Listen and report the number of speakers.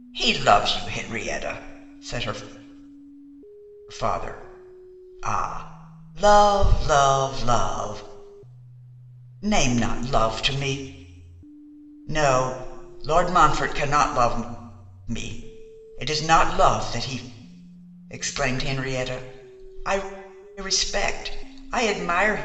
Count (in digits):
1